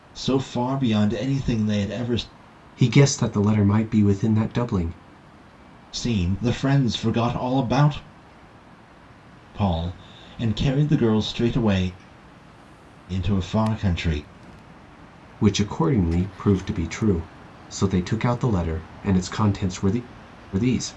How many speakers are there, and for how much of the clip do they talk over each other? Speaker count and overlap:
2, no overlap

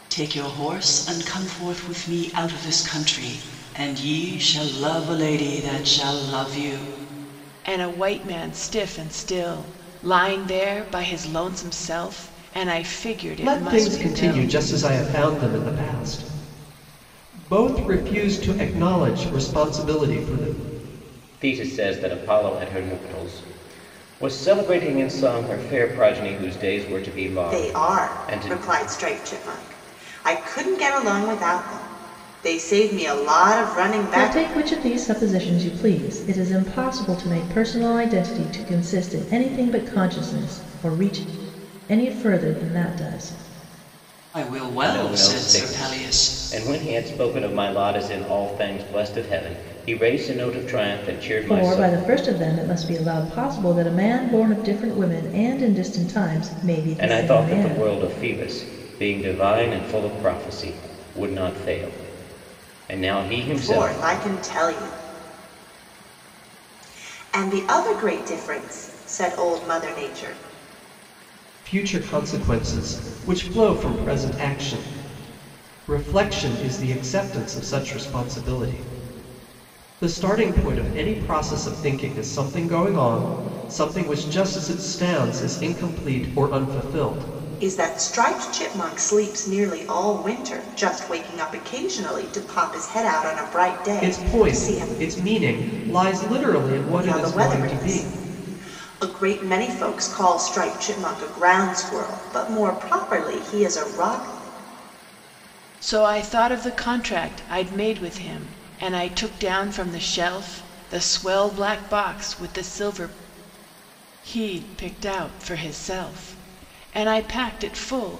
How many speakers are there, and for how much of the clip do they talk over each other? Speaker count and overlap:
6, about 7%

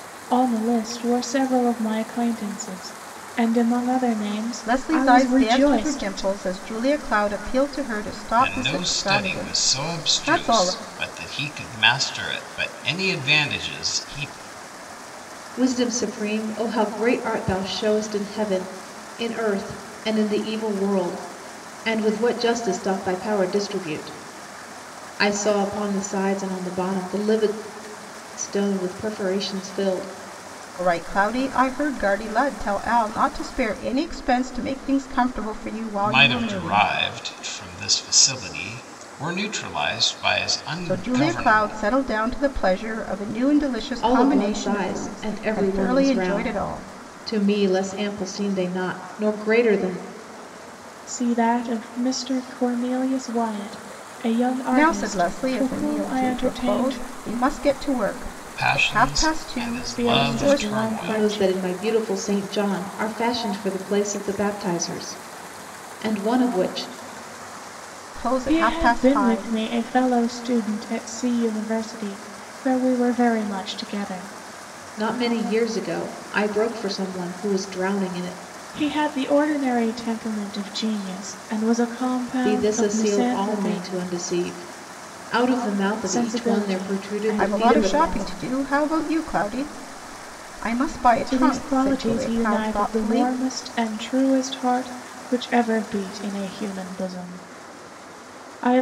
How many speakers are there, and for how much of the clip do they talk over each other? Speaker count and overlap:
4, about 22%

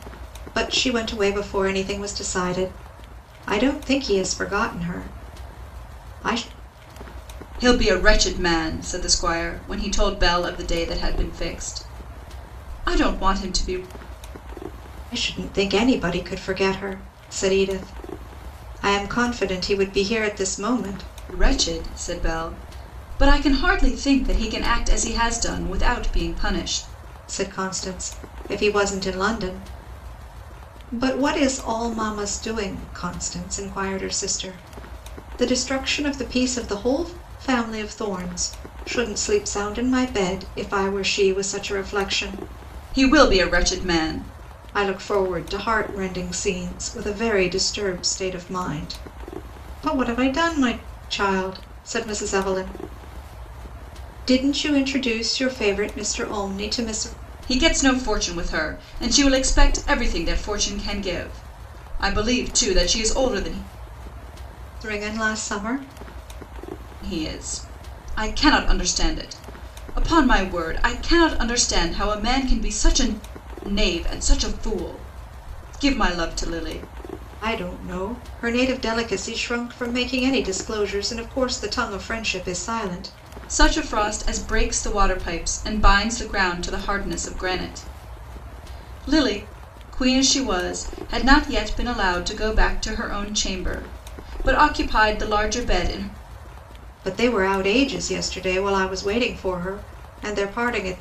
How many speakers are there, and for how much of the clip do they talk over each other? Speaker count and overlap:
2, no overlap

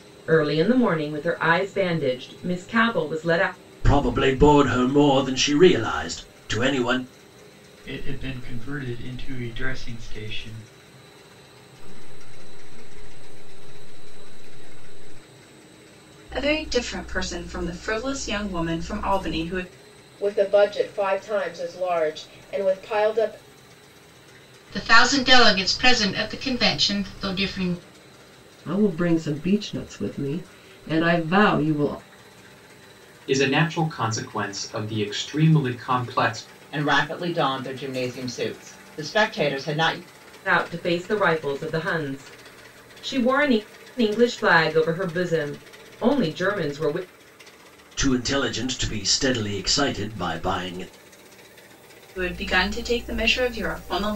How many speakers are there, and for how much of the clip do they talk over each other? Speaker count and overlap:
10, no overlap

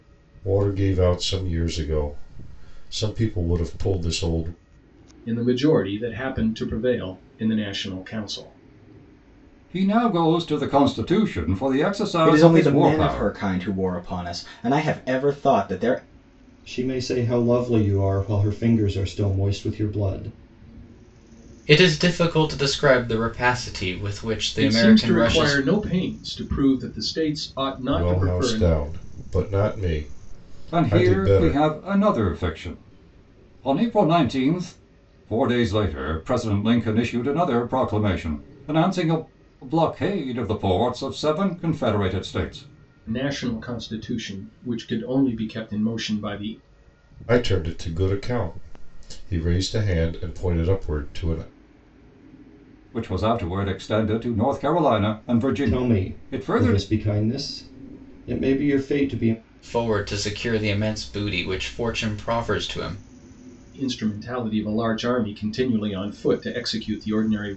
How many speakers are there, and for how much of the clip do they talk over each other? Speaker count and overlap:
6, about 8%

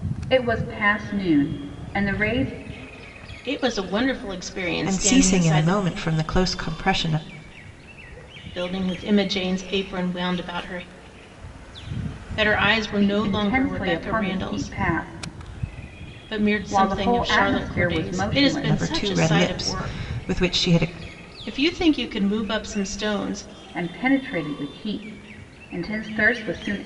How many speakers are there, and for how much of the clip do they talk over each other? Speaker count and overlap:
3, about 23%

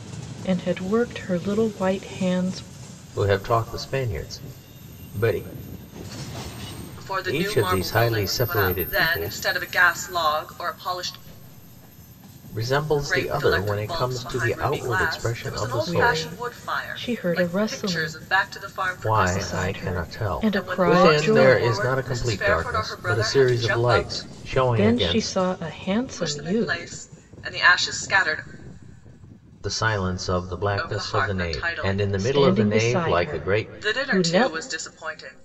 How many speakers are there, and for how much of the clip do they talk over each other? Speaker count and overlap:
3, about 51%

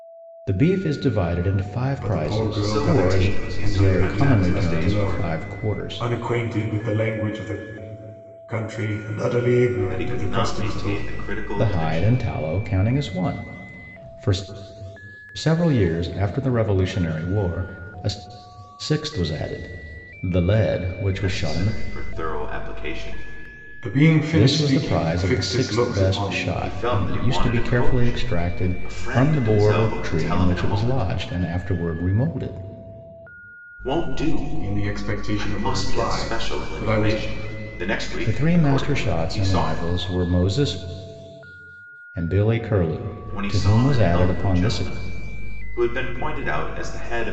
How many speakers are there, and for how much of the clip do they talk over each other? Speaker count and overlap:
3, about 41%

